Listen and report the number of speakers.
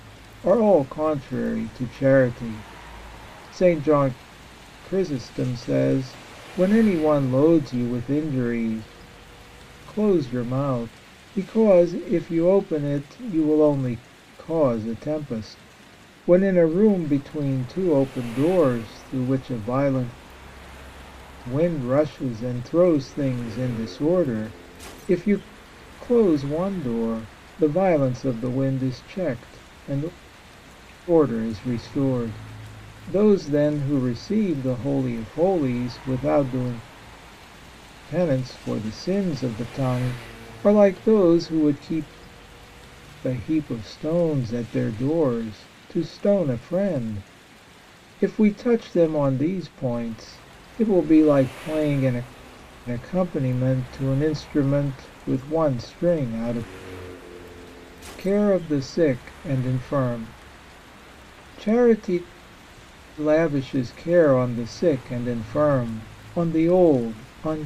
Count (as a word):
one